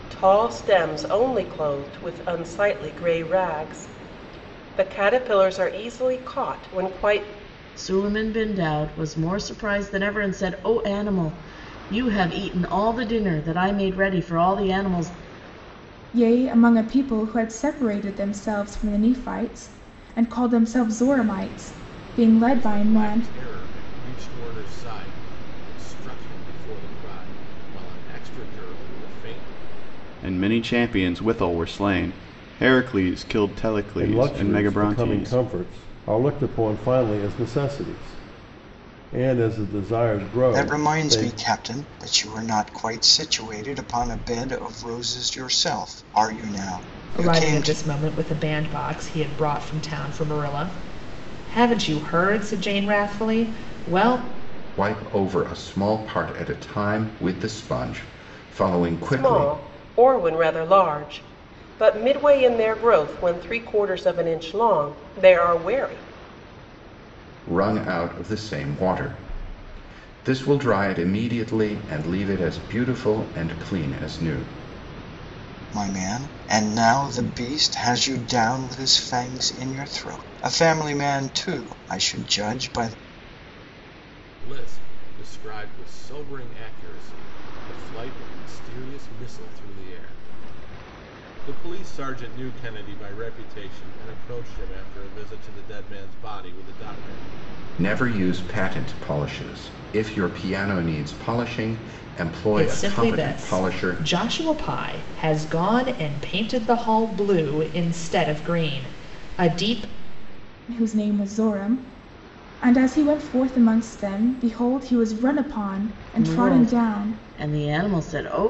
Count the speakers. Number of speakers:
9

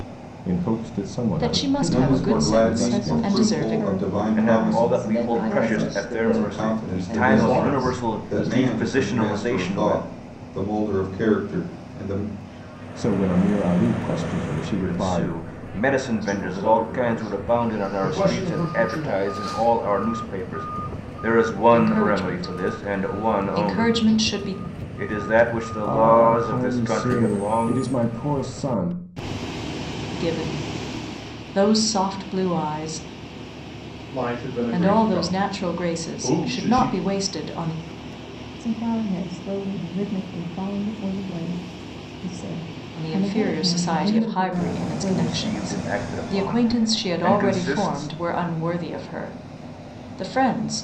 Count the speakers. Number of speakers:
7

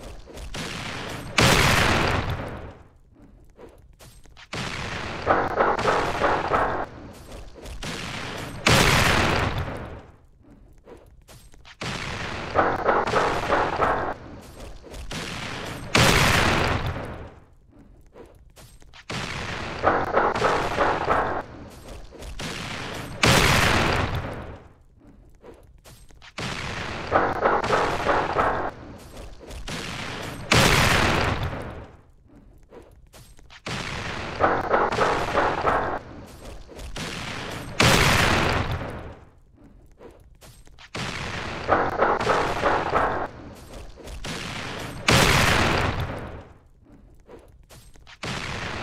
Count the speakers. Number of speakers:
0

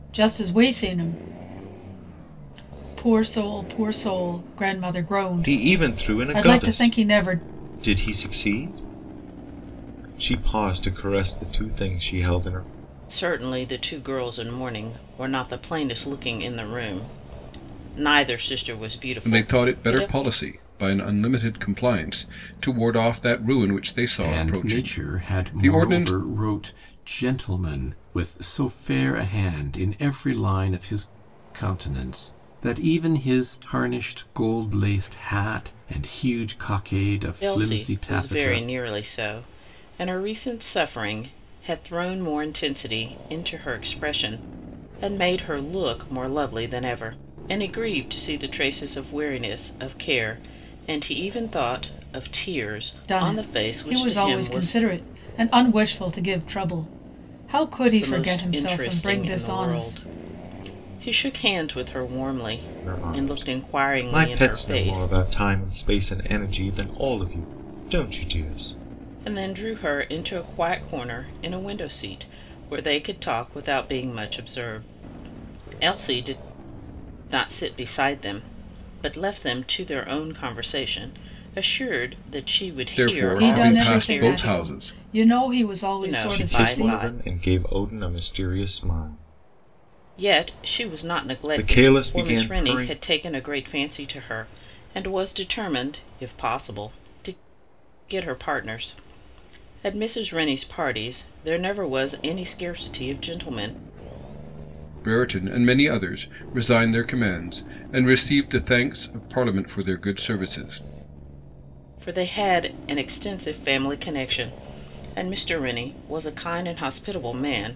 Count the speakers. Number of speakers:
5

